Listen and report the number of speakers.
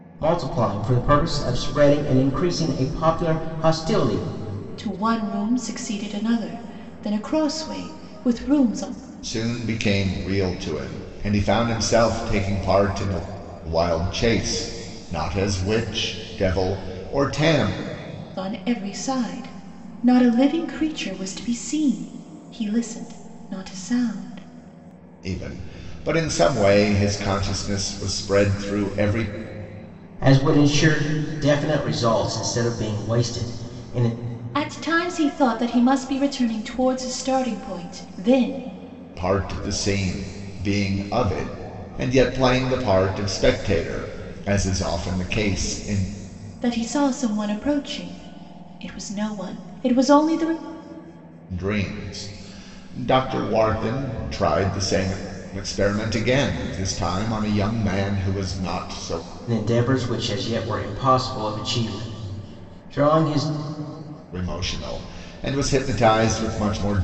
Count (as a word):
three